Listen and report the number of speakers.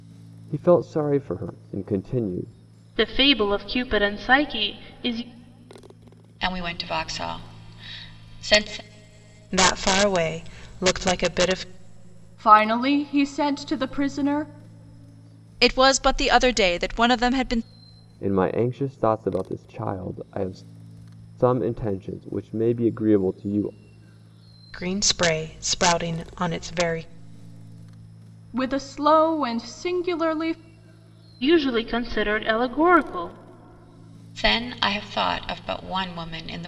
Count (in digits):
6